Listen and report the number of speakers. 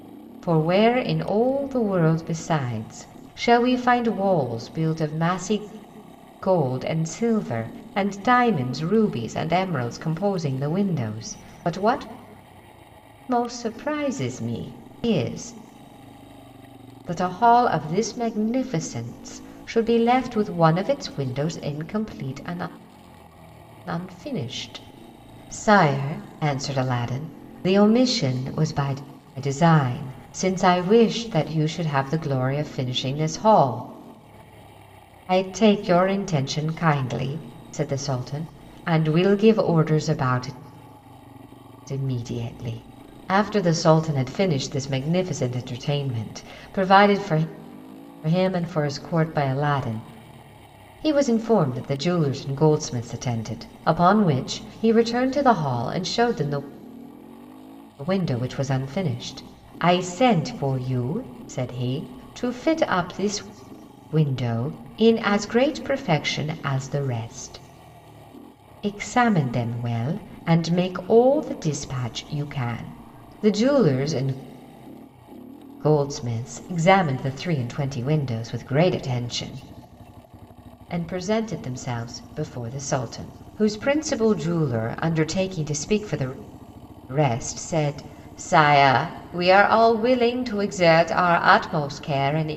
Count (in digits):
1